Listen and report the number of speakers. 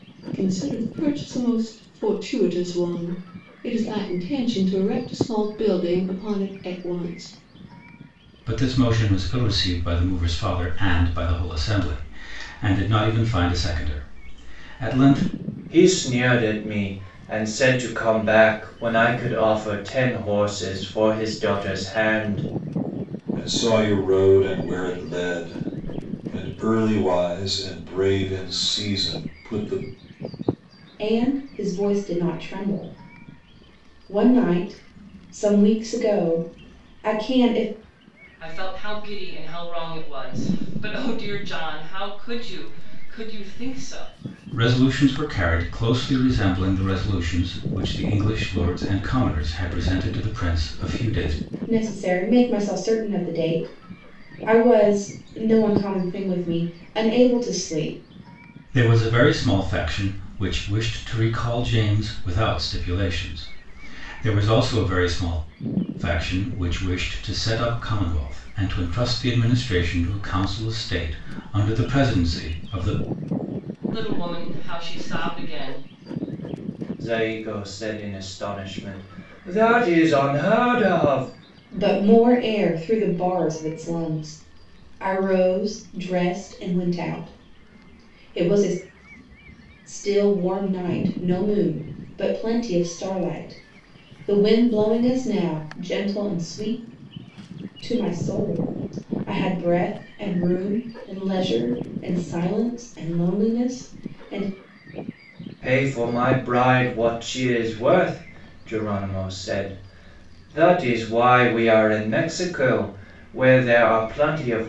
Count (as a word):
six